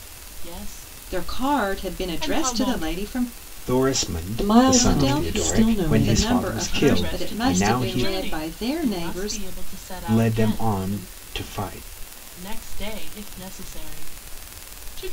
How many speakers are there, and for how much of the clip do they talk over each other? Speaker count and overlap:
4, about 51%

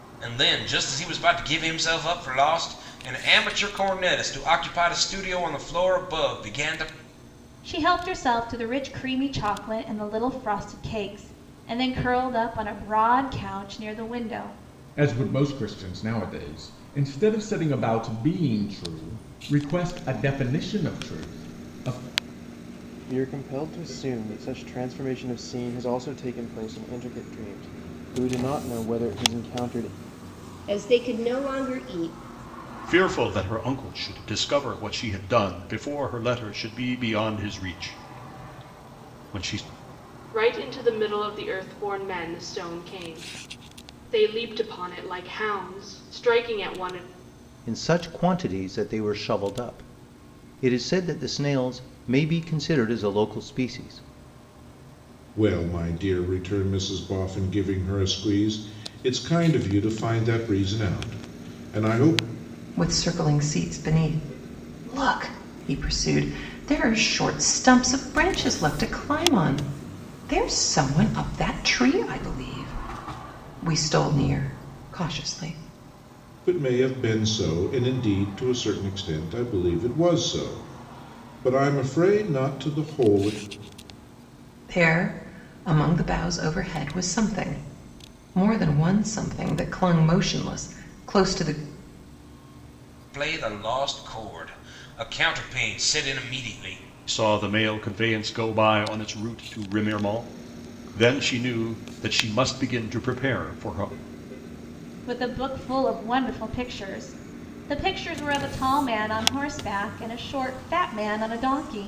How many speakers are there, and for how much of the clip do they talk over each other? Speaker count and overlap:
10, no overlap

